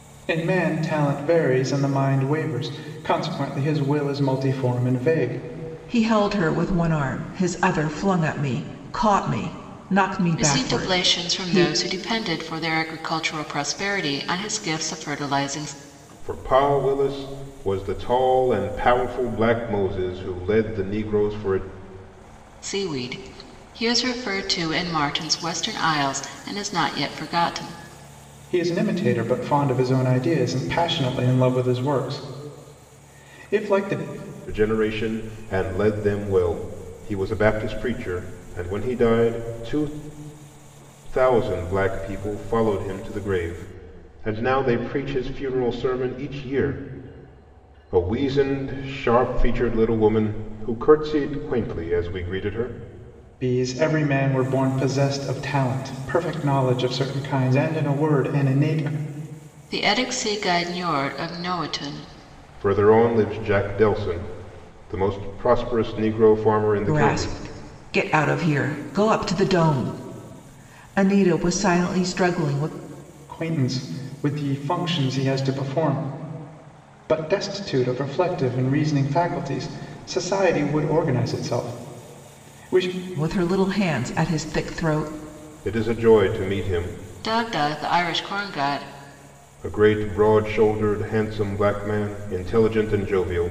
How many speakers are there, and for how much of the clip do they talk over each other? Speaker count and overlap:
4, about 2%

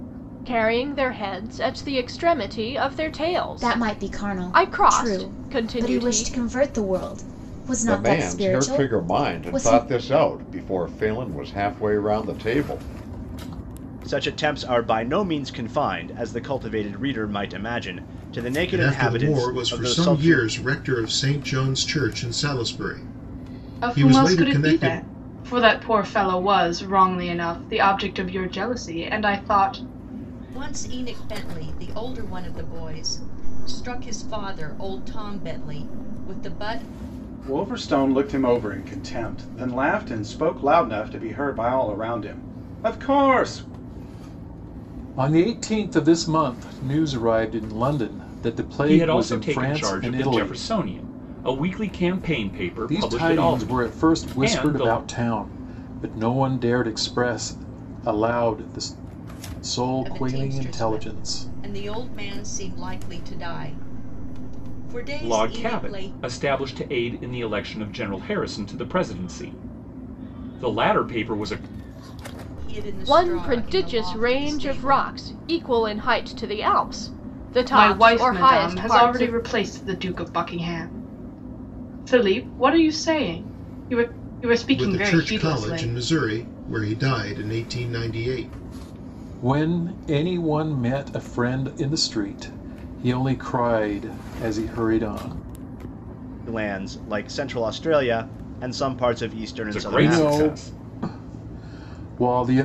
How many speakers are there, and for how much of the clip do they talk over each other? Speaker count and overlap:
10, about 19%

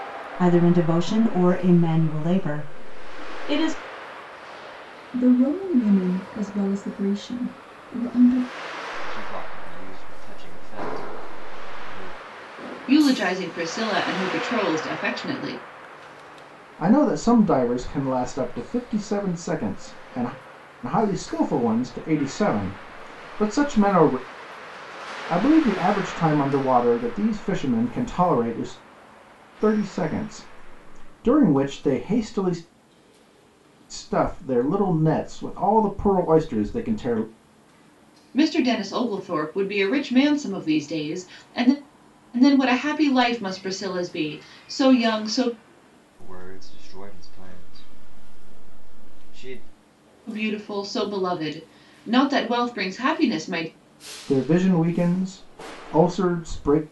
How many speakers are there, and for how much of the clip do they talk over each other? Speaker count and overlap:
5, no overlap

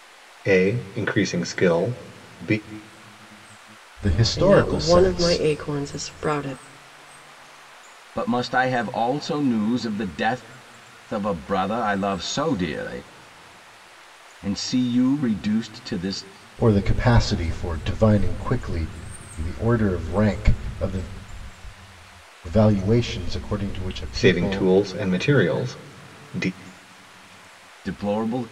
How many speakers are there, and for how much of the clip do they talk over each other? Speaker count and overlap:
4, about 6%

